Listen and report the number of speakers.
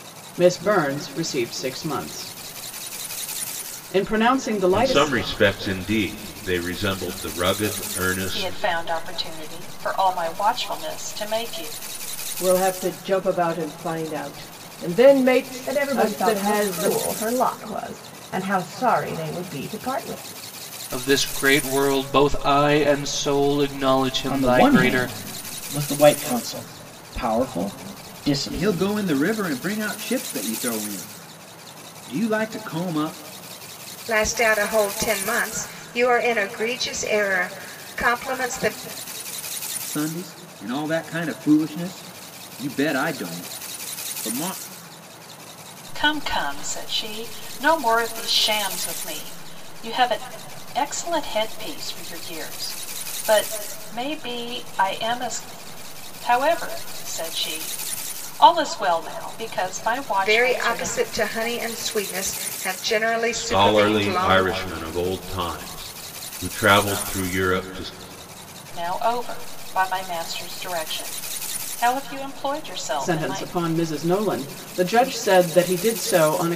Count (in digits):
9